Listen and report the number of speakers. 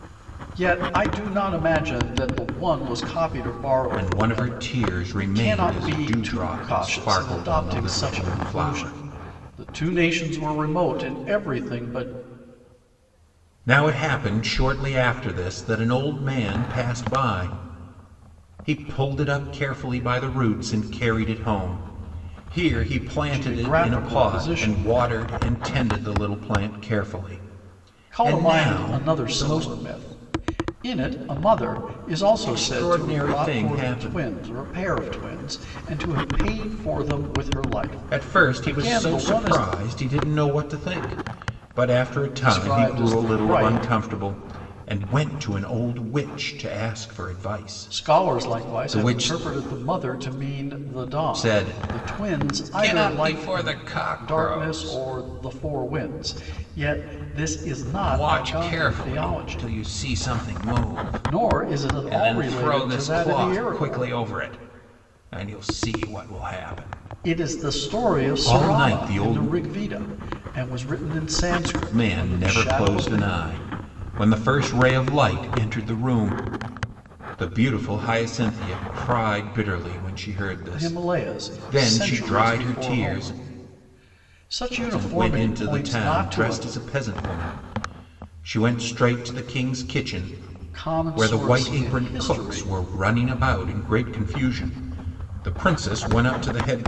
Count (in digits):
2